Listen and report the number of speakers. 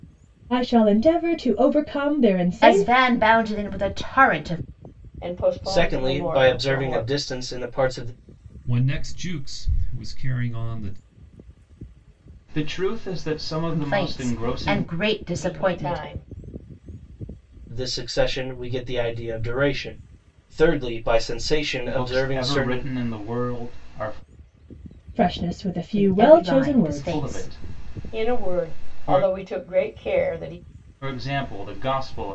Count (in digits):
6